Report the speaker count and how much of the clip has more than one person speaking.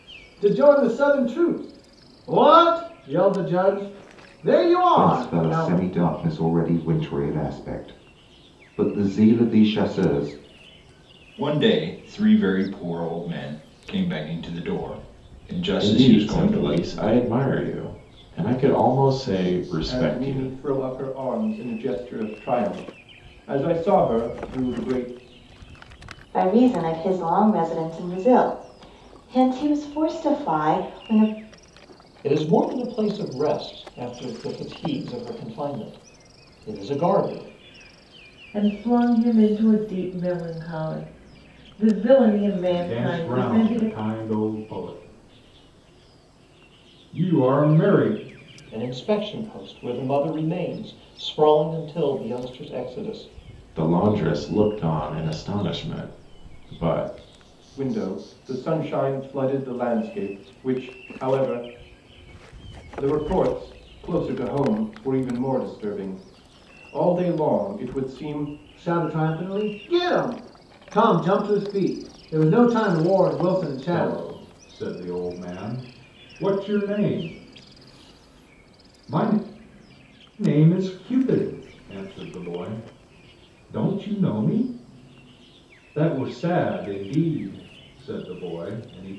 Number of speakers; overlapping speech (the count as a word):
nine, about 5%